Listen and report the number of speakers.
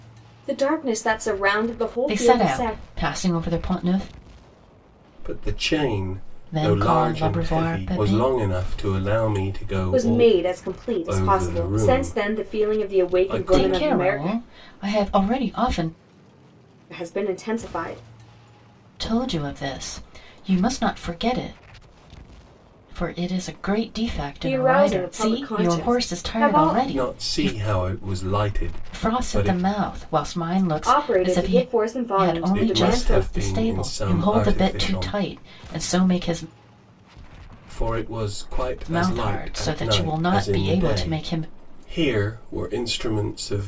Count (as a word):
three